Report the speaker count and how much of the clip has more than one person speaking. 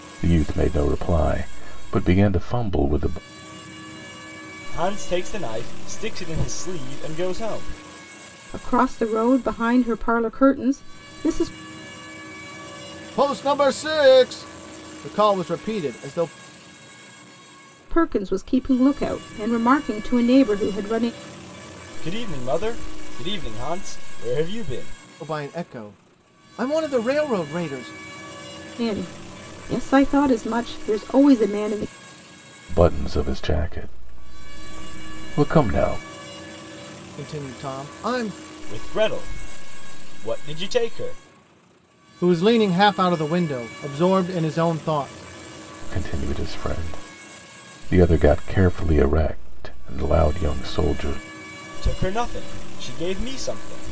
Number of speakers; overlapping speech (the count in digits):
4, no overlap